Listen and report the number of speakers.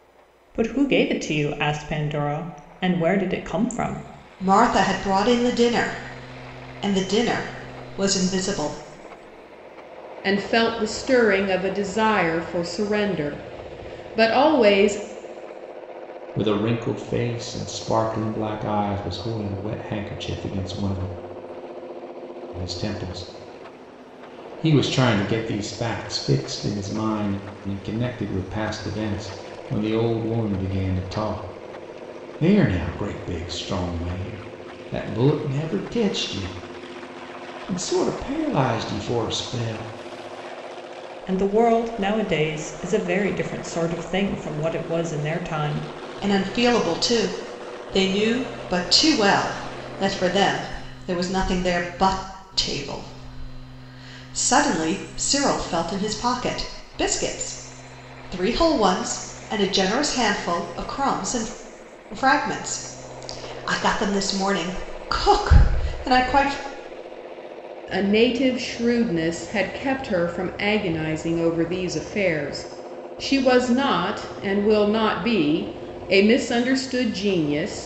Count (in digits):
4